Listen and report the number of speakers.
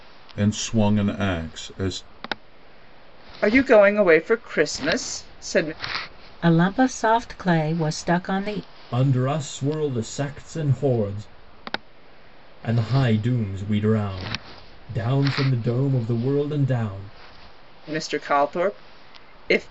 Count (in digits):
4